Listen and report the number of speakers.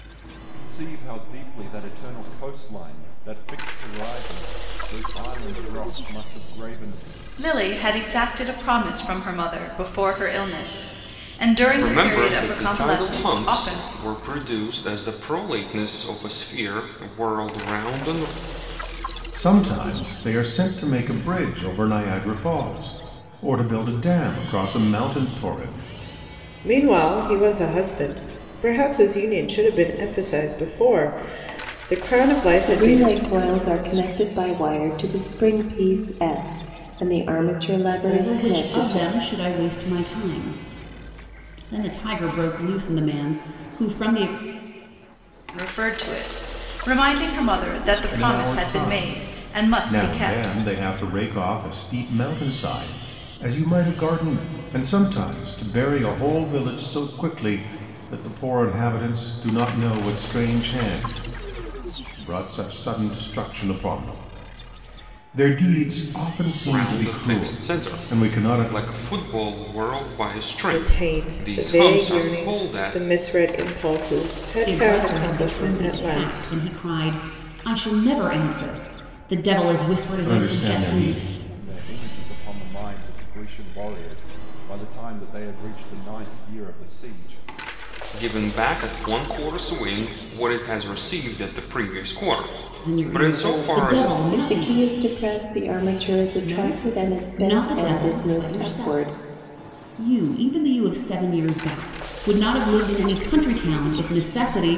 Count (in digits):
7